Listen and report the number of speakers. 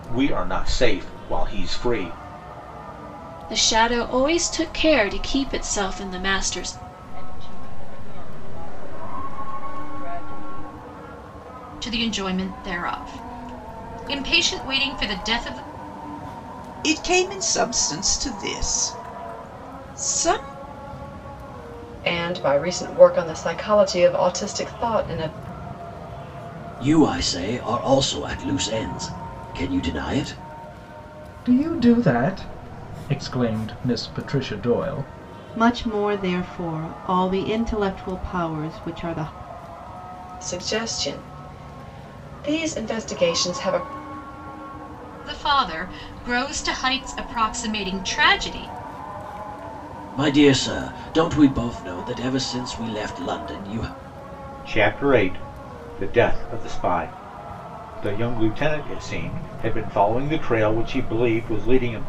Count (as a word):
nine